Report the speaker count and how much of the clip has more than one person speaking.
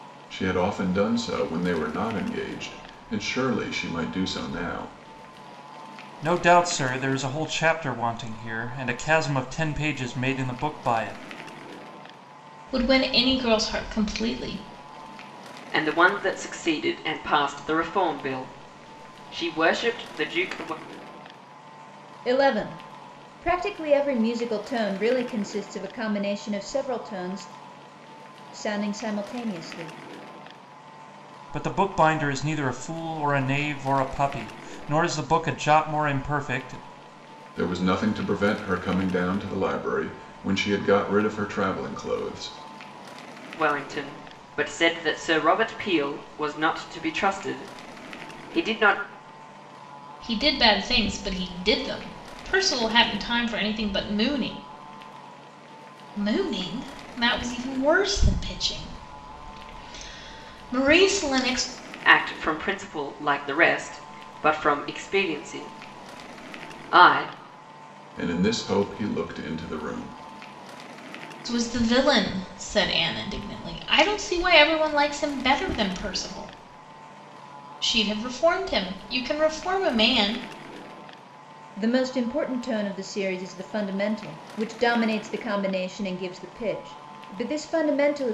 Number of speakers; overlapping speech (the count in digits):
5, no overlap